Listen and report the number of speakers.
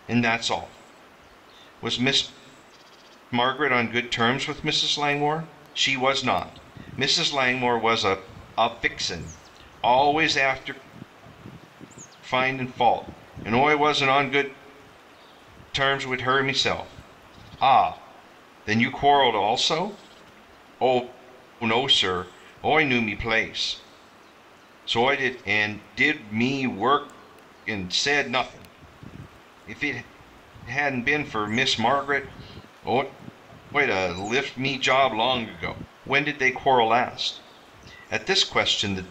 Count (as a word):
one